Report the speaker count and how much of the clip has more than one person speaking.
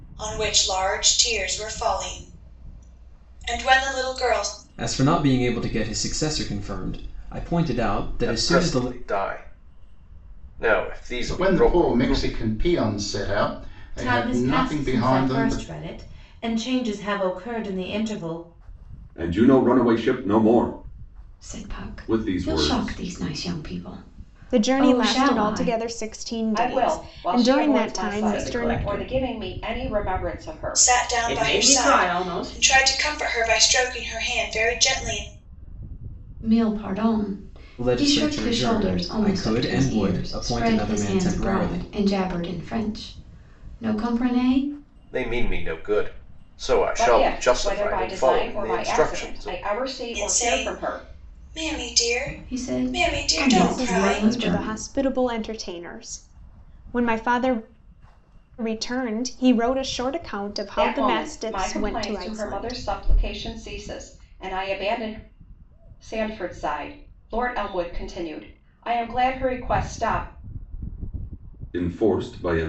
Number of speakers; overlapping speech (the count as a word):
ten, about 34%